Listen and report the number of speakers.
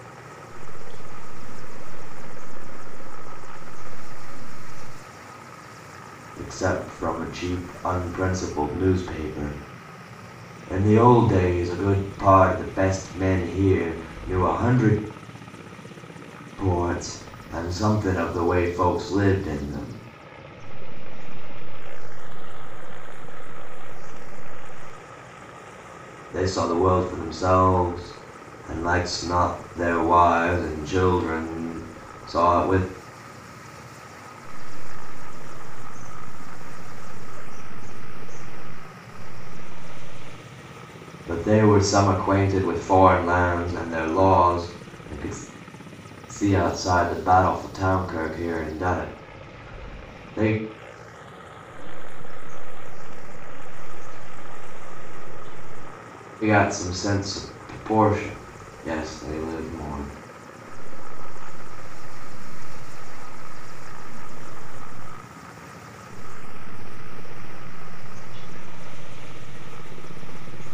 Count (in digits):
2